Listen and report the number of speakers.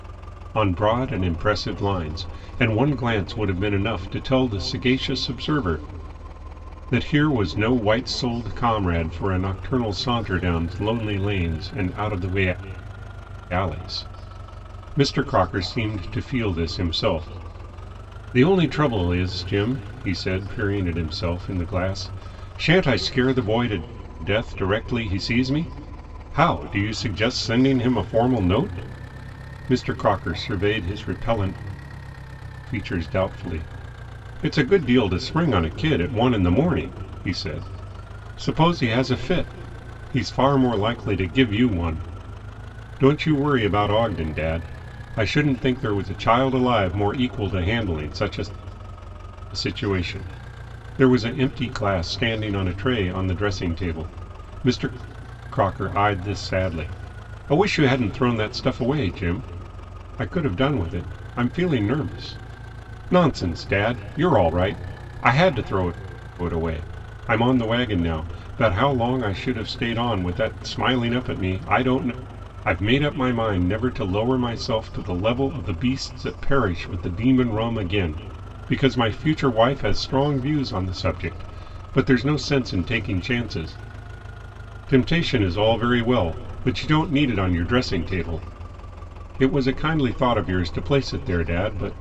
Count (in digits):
1